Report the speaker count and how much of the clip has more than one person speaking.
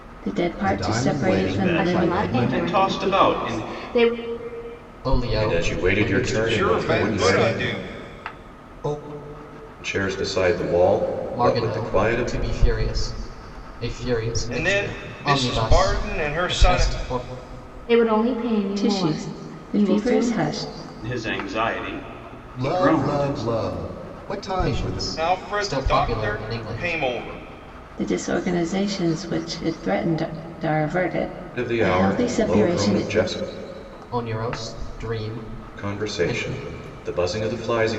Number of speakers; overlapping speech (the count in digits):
7, about 42%